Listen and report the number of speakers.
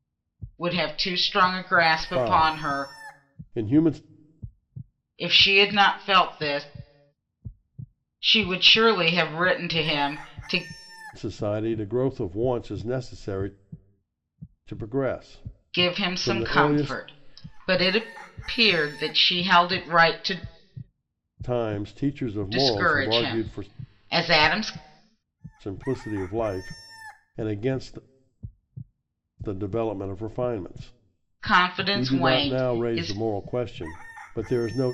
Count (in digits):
2